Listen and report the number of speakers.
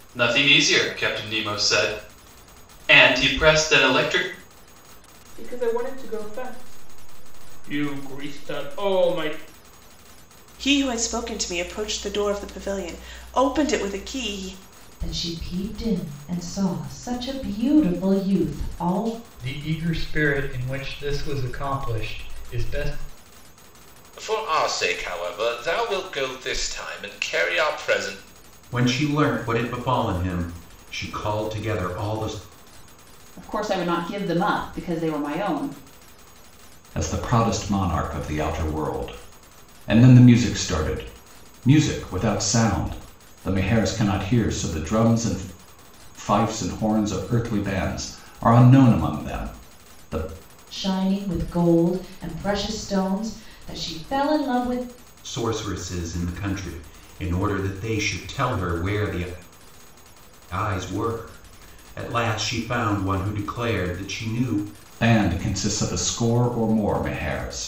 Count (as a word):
nine